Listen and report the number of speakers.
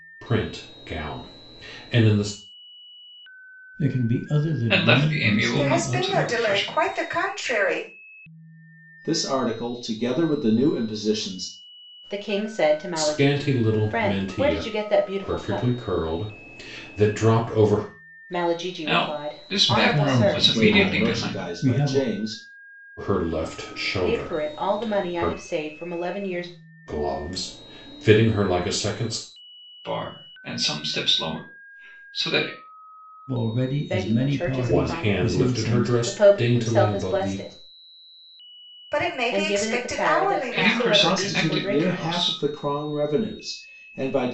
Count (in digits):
6